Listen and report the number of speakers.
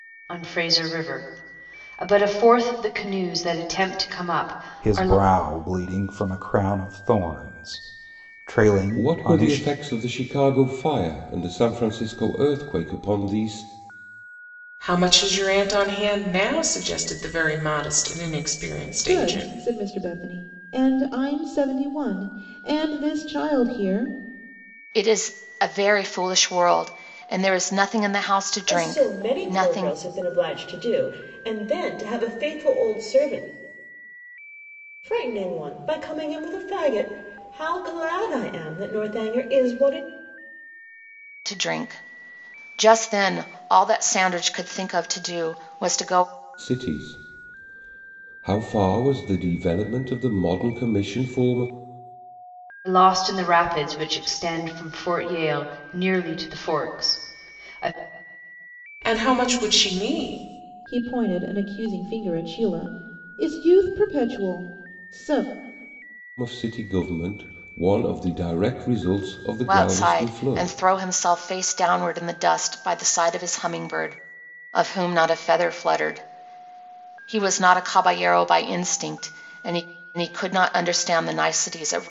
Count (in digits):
7